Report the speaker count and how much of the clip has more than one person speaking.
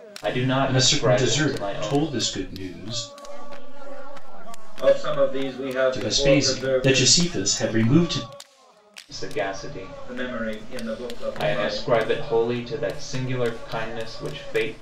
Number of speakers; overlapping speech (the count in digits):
4, about 36%